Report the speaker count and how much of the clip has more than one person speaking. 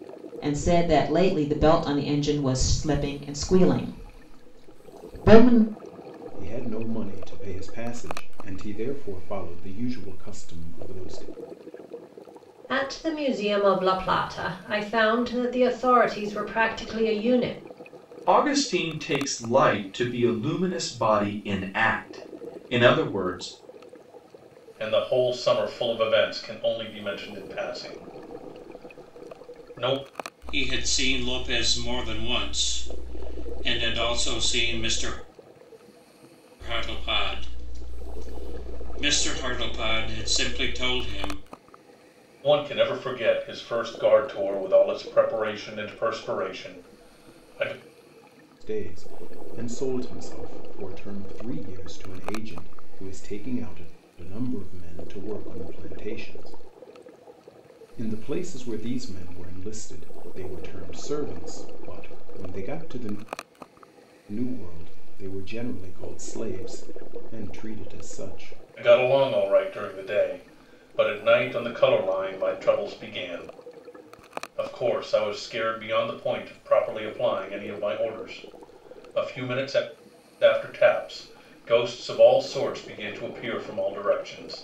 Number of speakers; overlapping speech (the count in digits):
6, no overlap